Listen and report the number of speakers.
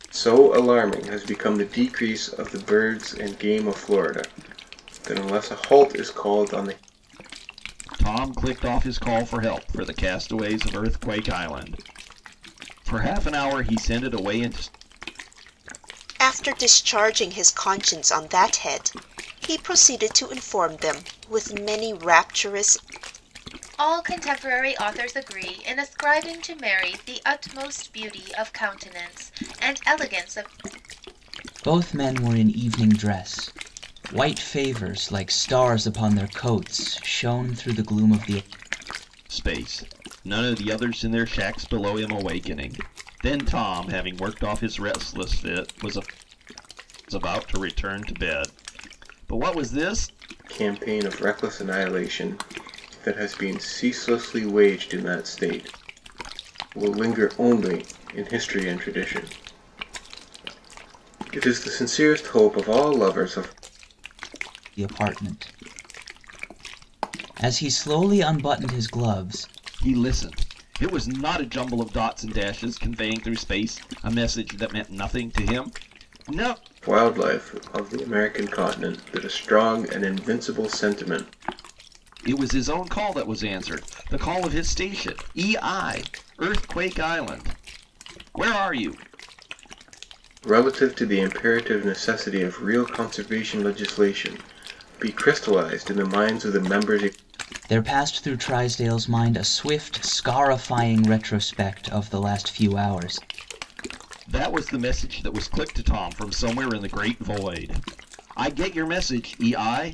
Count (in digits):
5